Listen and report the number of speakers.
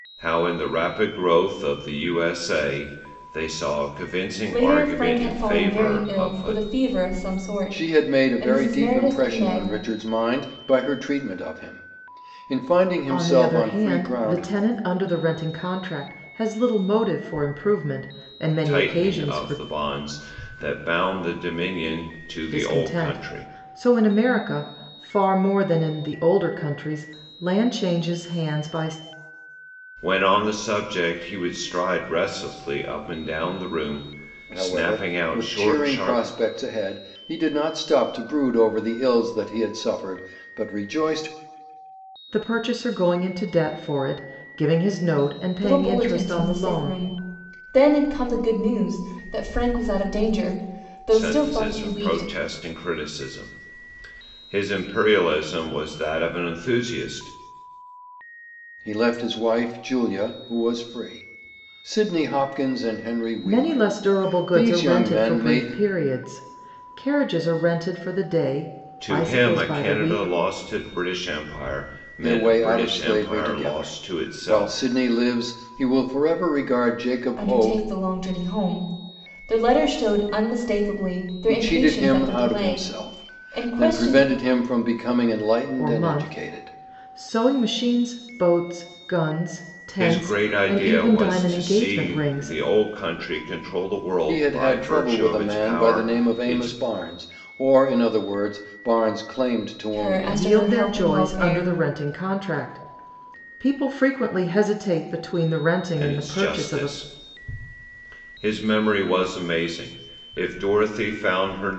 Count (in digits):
4